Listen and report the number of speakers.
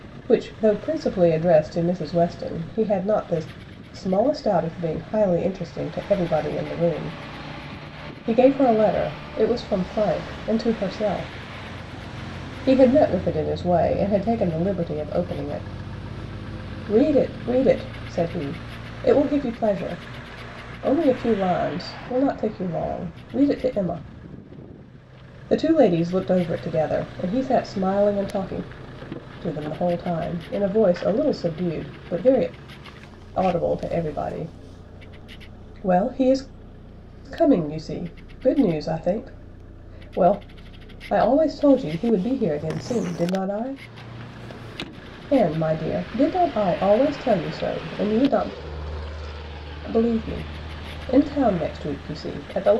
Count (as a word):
one